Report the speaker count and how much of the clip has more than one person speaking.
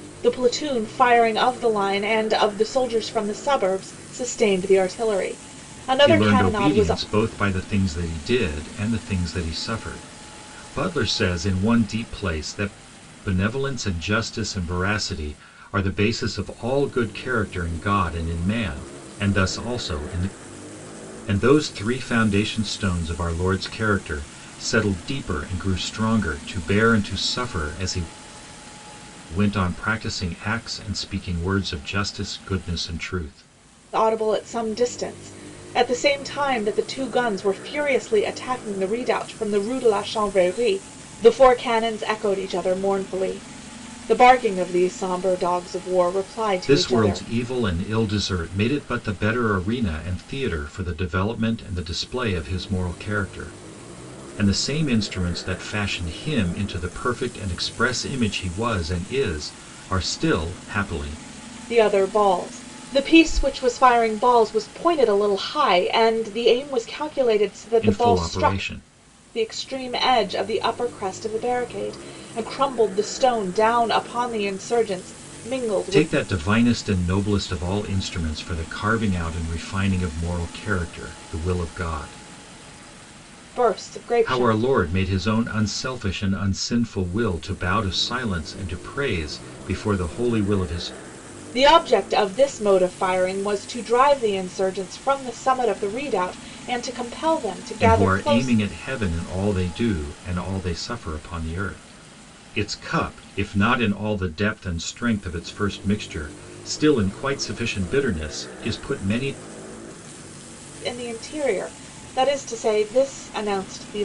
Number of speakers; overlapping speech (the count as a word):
two, about 4%